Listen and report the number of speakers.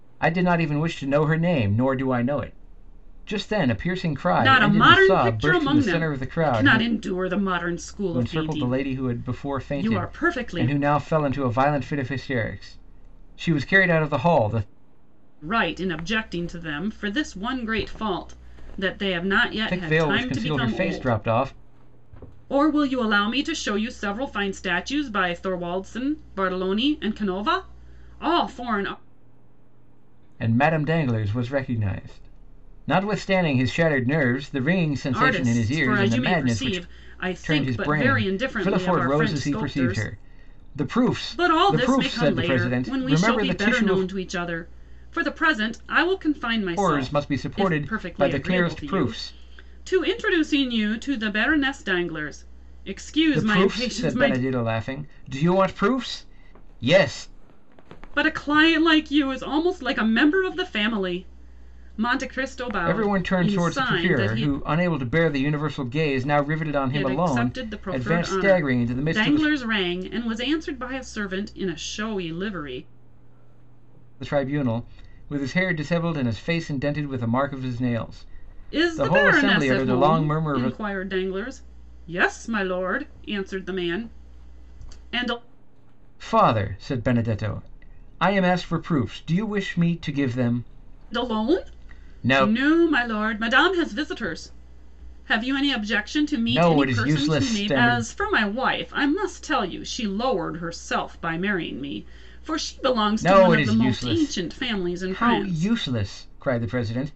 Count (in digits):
2